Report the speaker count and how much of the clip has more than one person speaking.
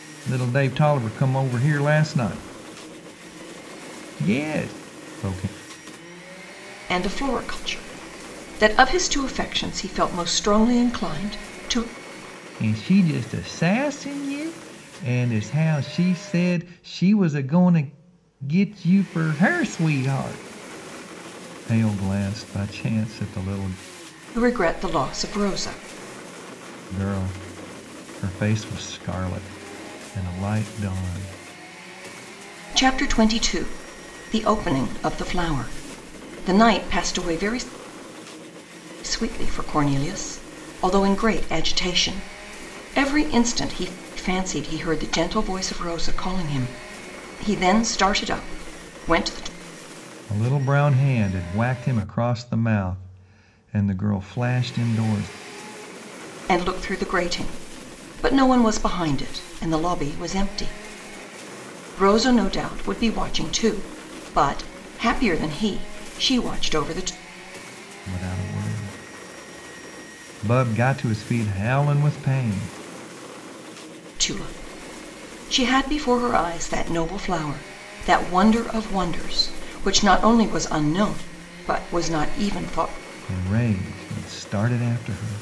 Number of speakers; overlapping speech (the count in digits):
2, no overlap